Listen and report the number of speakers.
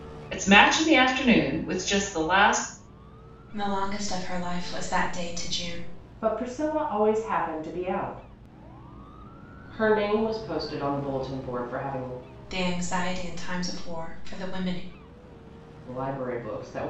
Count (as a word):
three